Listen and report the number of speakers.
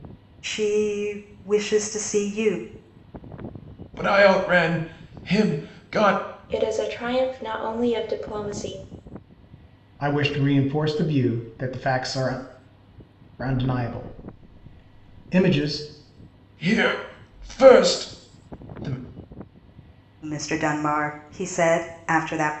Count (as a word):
four